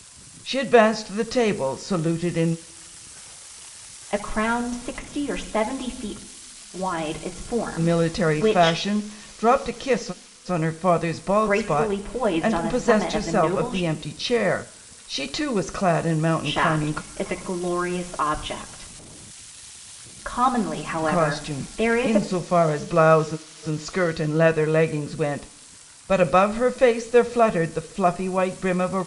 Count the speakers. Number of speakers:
2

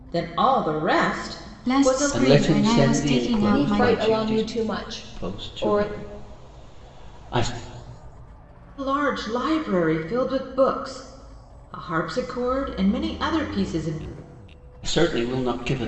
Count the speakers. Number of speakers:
4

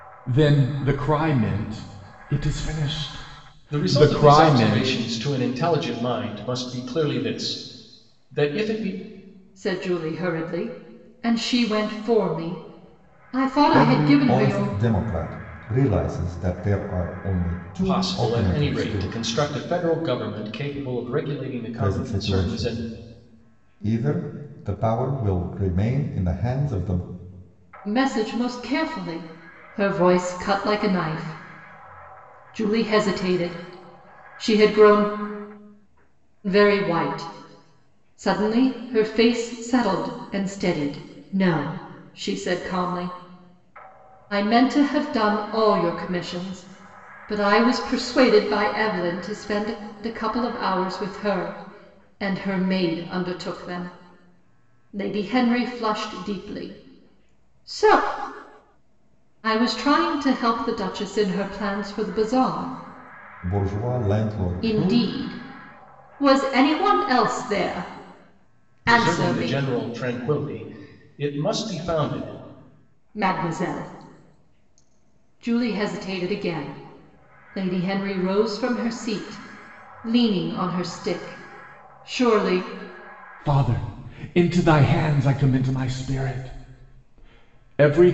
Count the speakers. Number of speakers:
4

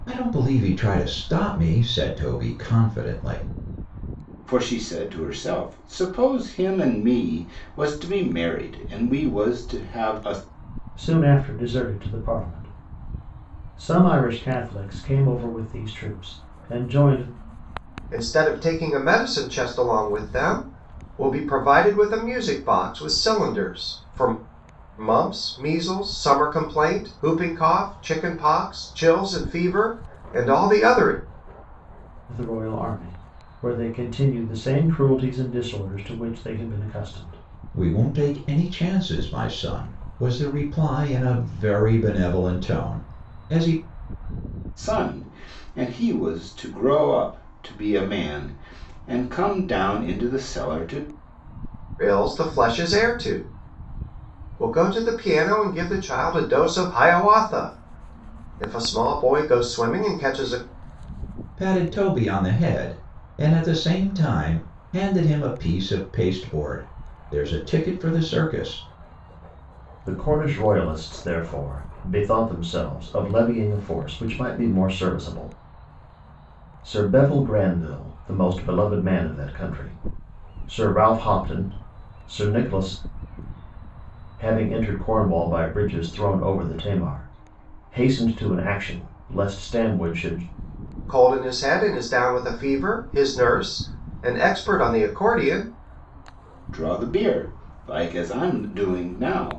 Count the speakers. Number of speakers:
4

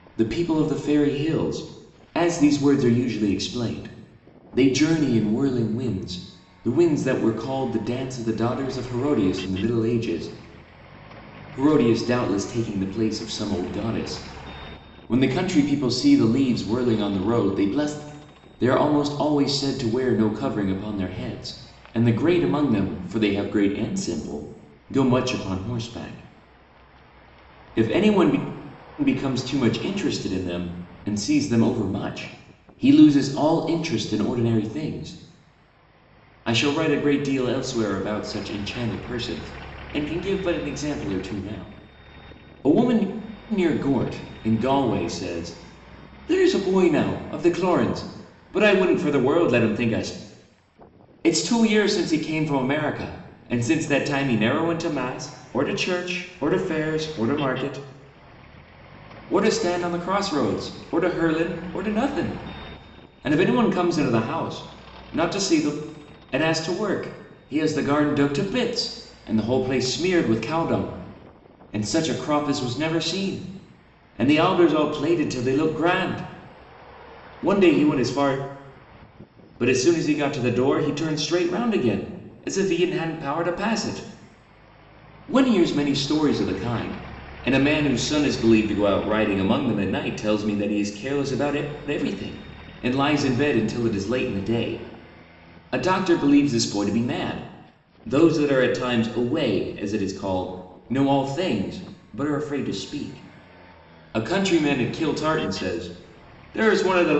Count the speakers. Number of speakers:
1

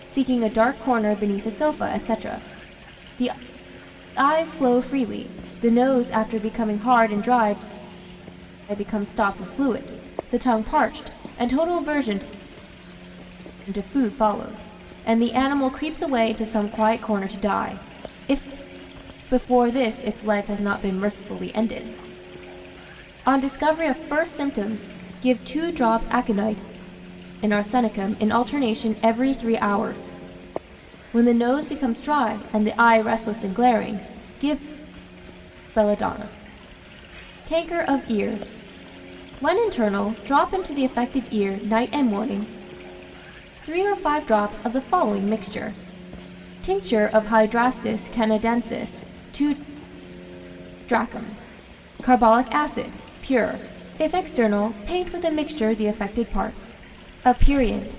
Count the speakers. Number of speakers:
1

